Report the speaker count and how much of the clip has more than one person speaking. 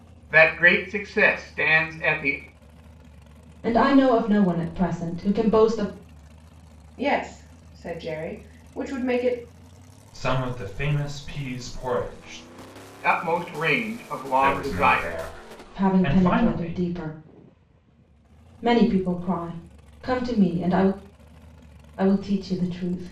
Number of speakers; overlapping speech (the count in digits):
4, about 9%